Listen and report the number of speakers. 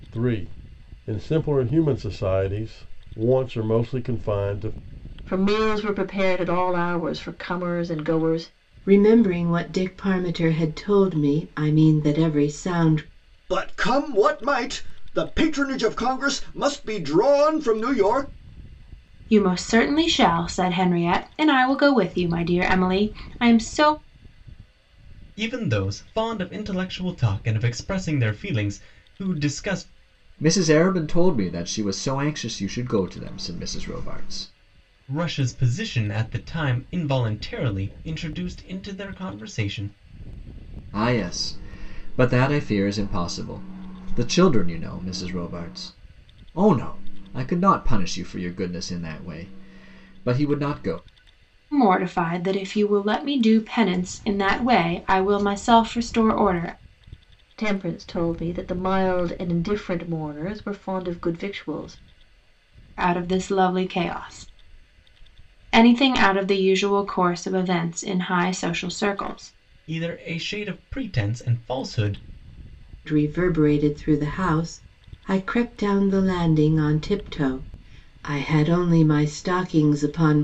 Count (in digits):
7